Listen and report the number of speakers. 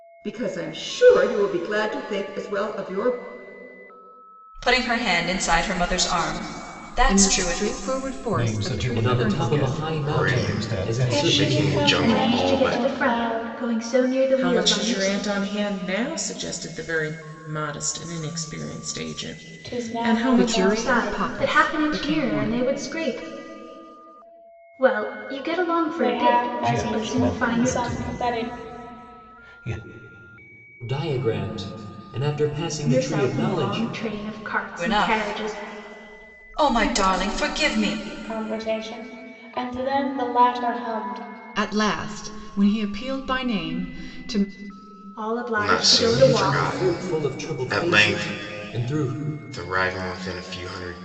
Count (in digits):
9